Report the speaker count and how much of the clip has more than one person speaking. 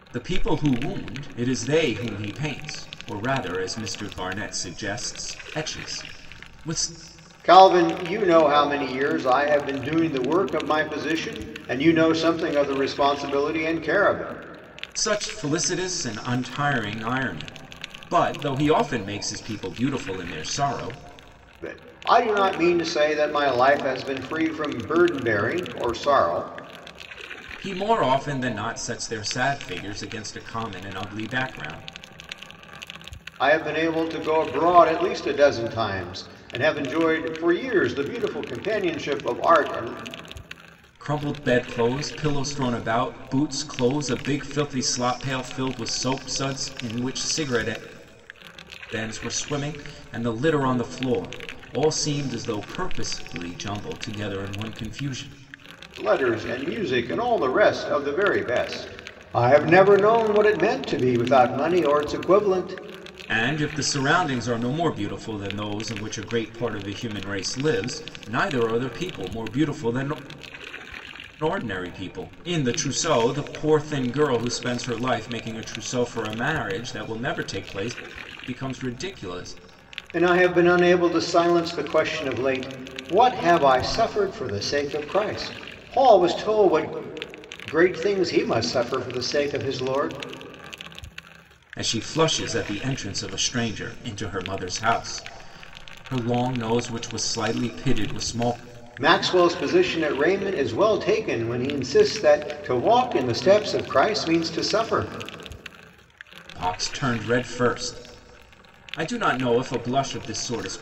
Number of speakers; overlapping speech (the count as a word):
two, no overlap